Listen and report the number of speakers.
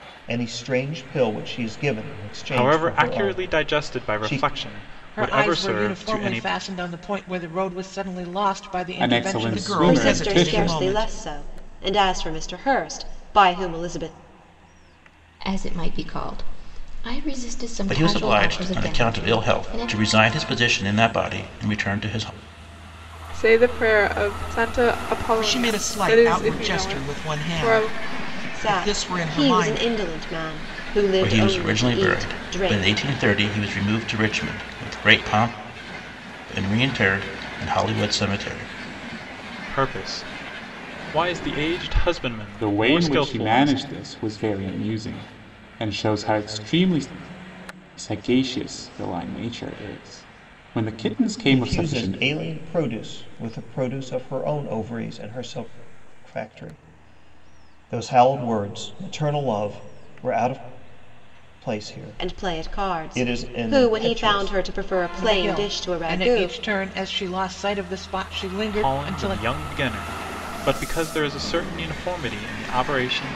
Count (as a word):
nine